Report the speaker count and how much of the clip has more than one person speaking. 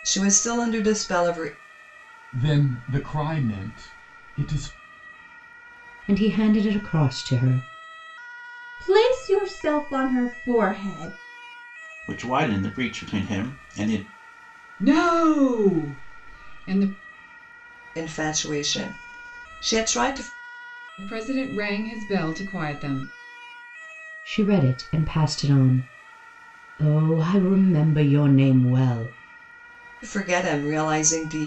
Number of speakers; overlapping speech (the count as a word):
six, no overlap